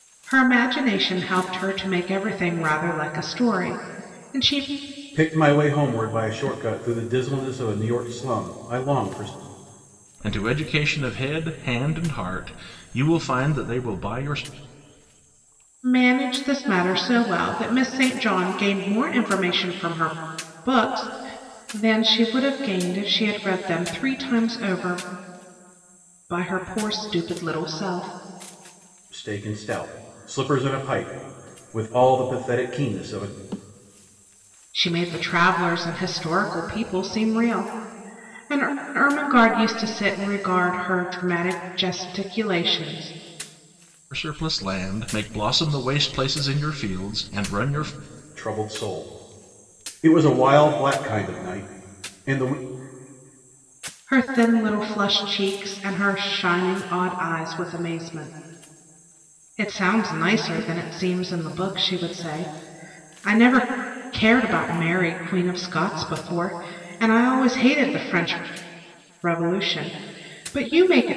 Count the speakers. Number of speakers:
3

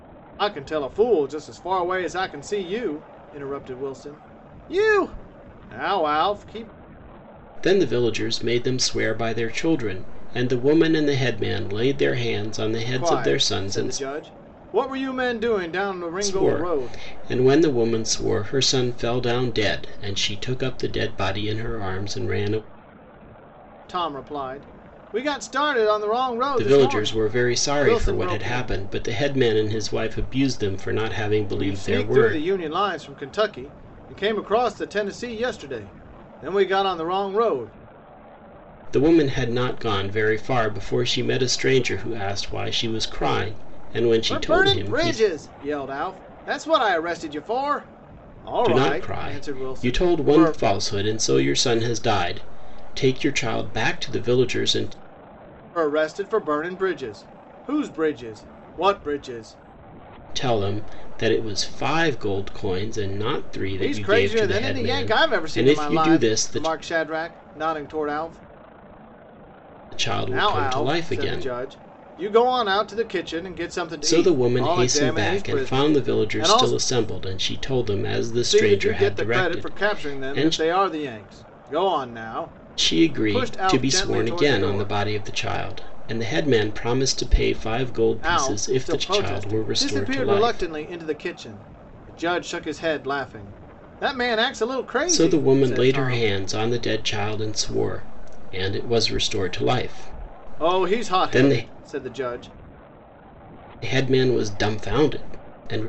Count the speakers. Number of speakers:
2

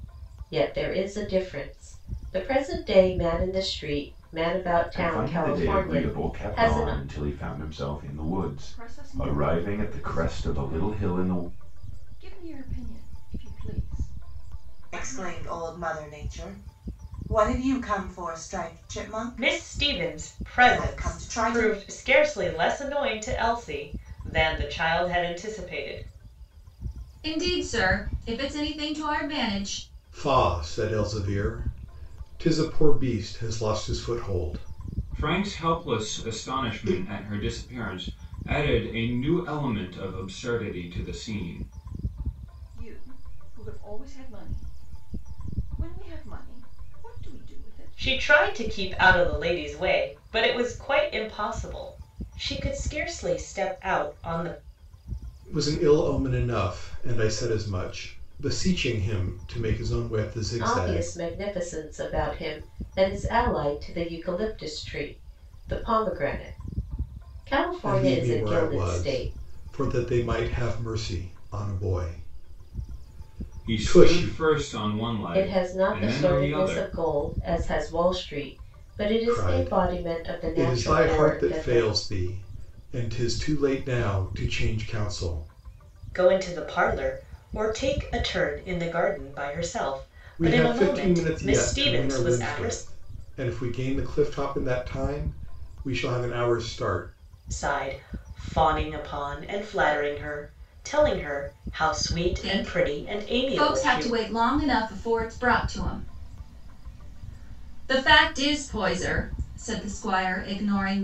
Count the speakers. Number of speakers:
8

